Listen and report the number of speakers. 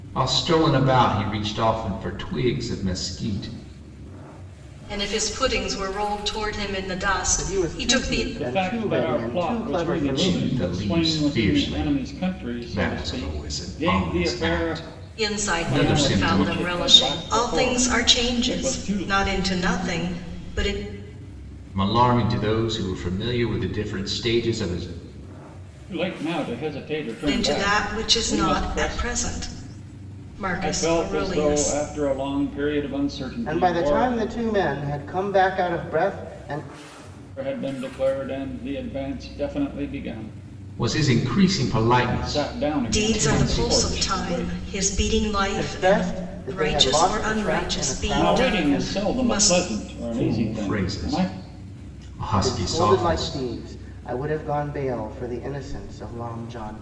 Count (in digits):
4